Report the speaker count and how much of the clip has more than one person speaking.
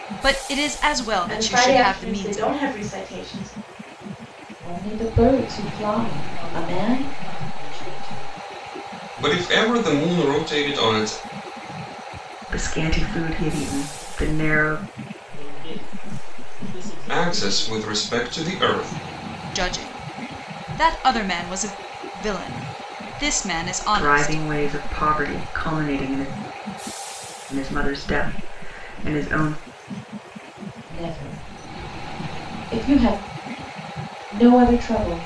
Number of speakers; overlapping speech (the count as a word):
six, about 10%